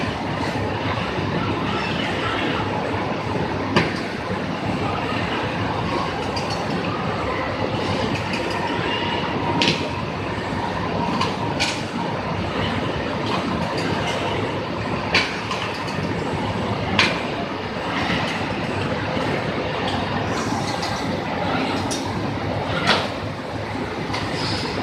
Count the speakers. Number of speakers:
0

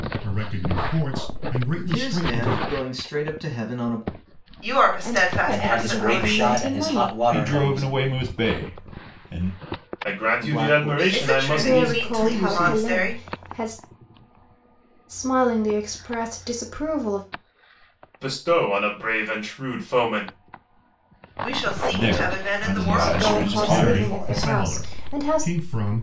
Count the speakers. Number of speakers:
7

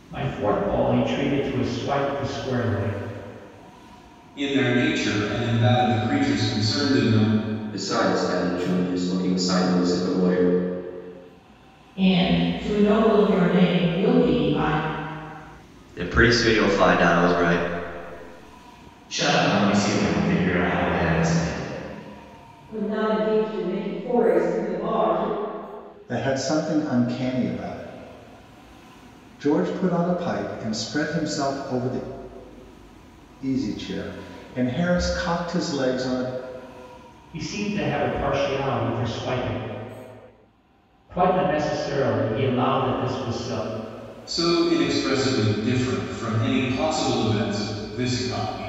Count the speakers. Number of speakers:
8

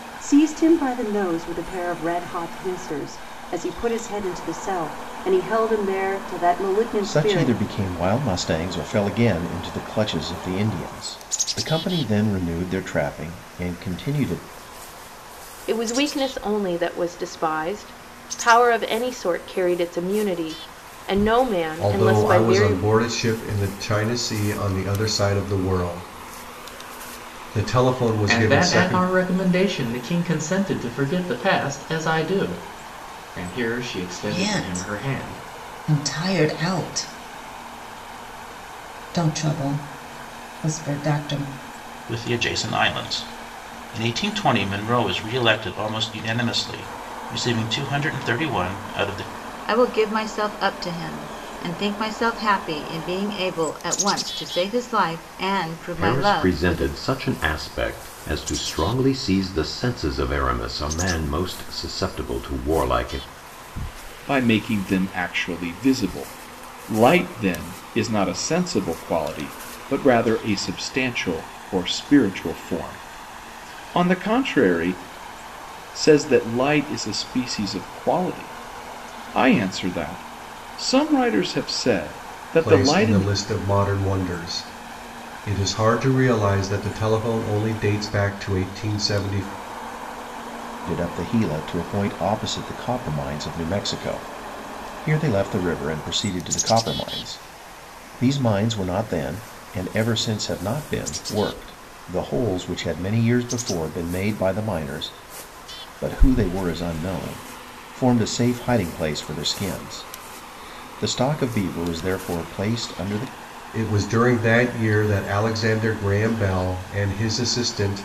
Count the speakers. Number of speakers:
10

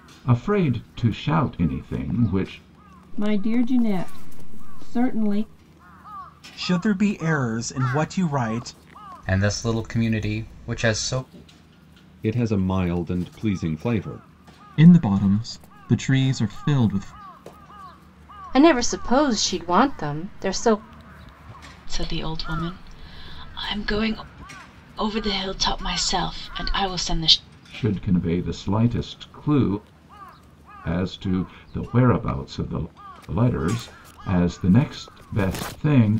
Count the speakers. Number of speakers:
8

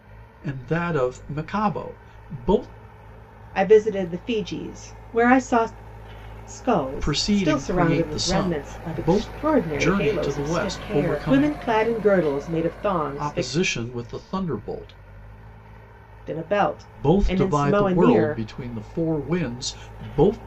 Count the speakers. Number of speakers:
2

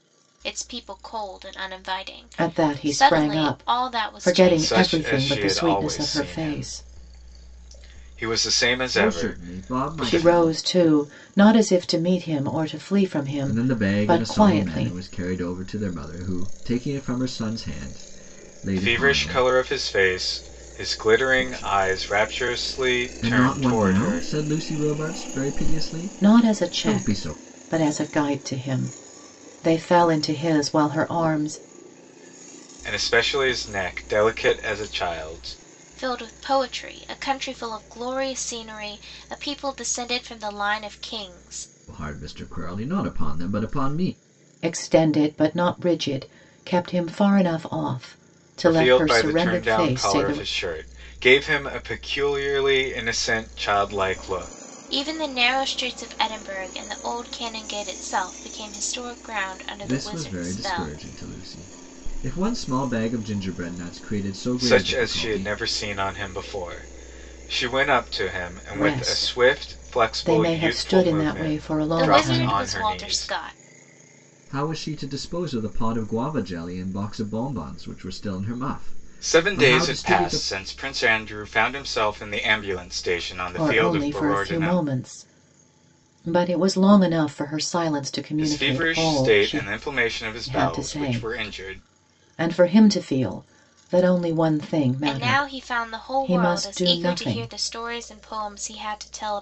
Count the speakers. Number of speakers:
4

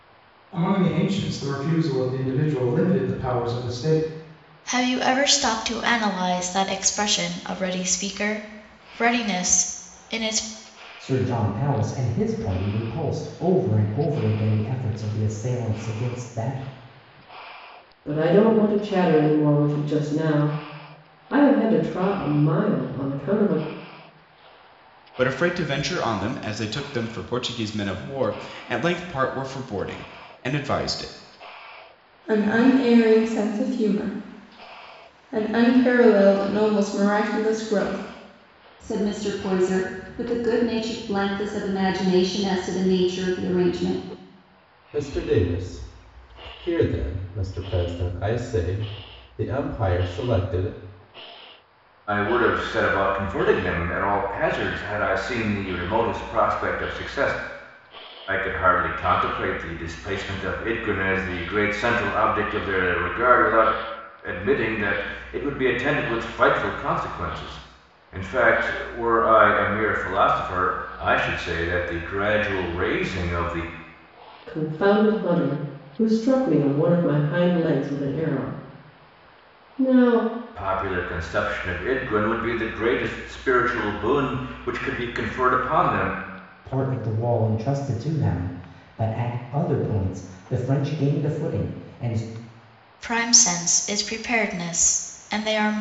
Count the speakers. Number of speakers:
9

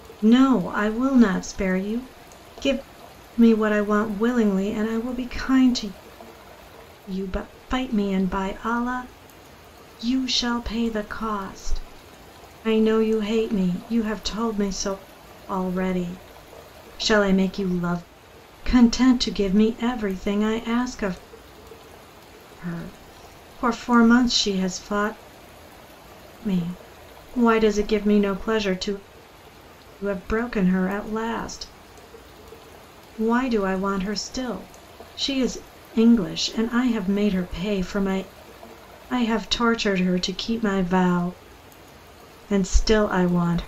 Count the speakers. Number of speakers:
1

